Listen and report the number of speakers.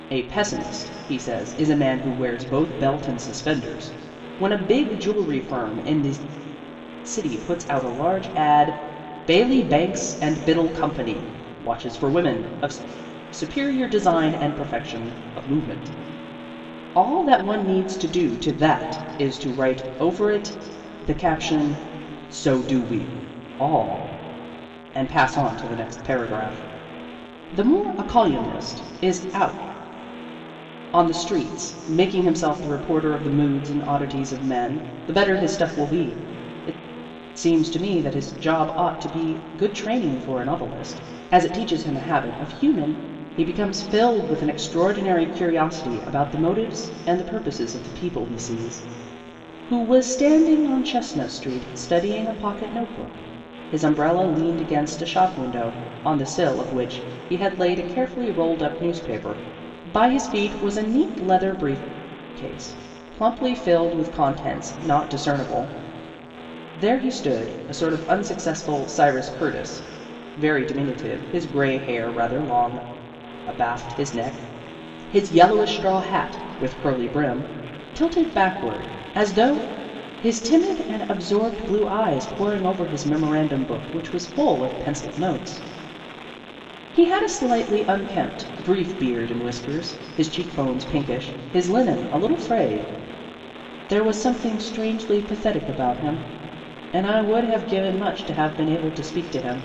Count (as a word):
one